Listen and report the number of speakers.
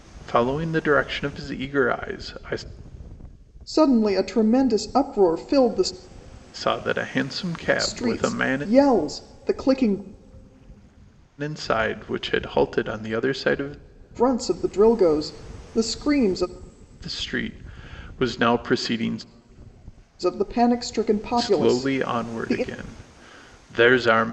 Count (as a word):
two